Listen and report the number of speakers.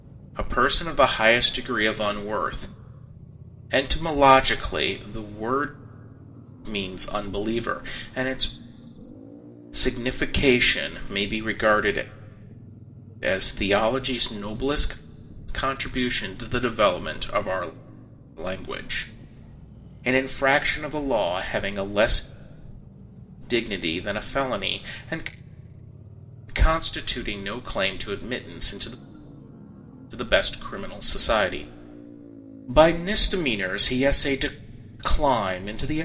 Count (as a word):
one